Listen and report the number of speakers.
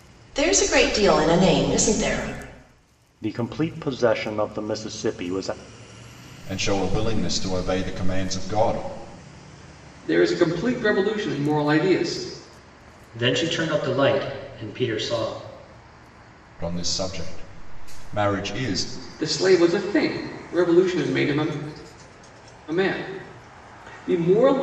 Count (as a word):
five